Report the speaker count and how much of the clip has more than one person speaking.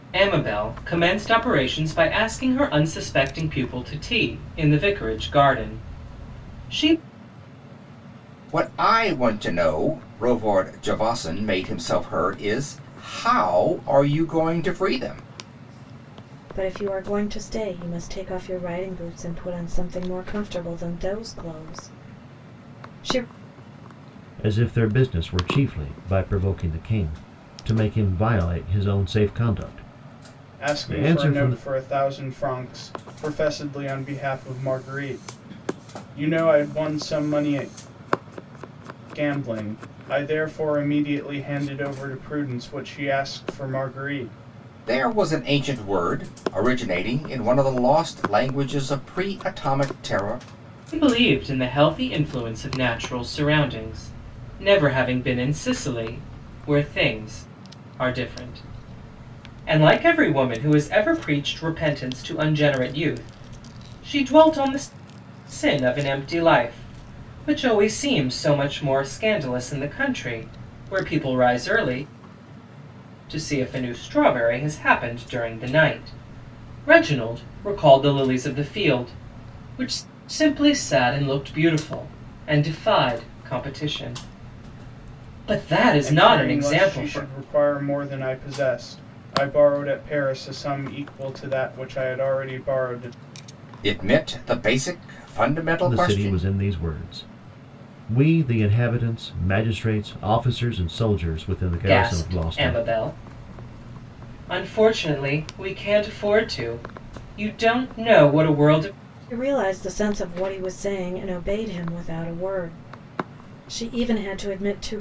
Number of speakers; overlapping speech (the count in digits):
5, about 3%